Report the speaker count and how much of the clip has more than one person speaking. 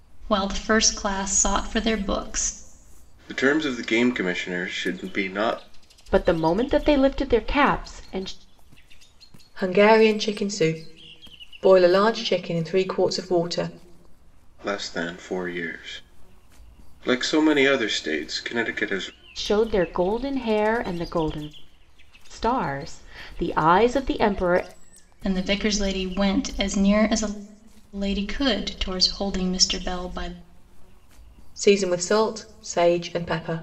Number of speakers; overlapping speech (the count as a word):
four, no overlap